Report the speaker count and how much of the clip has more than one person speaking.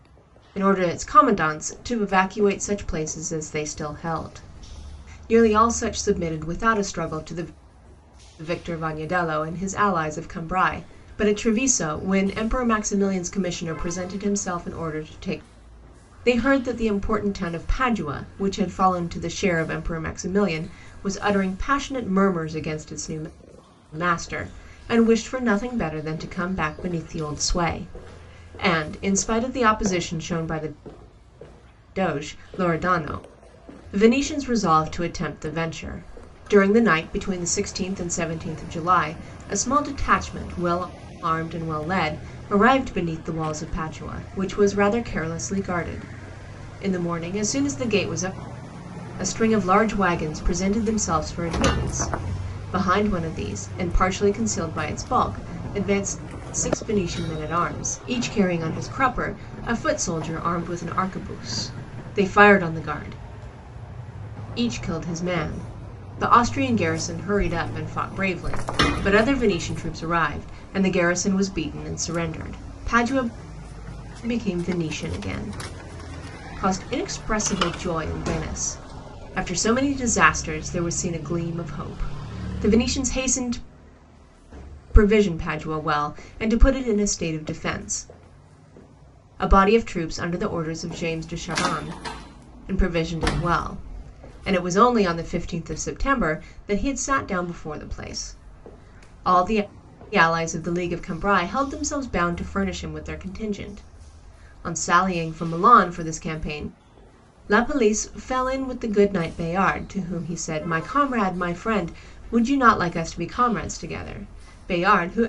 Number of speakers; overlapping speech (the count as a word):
one, no overlap